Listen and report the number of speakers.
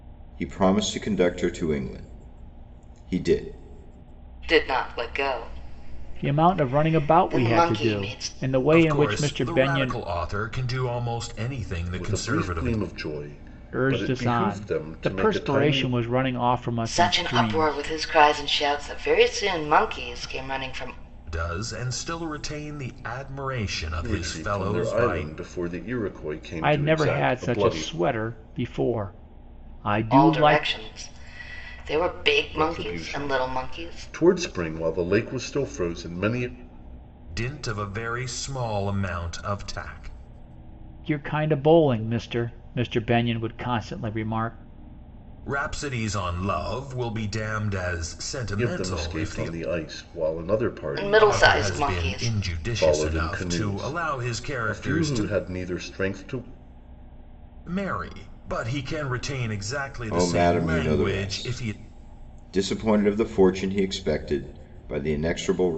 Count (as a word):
five